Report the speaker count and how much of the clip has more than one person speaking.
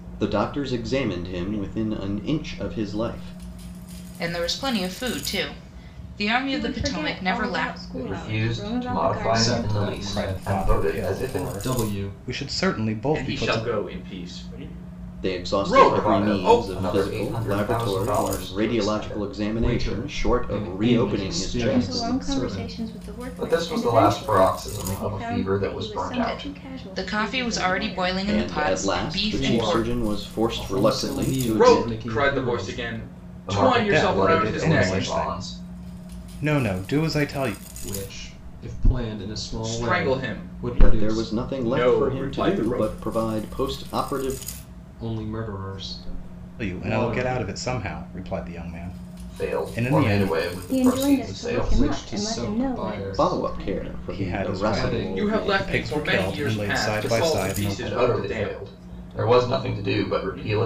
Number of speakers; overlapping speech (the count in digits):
7, about 63%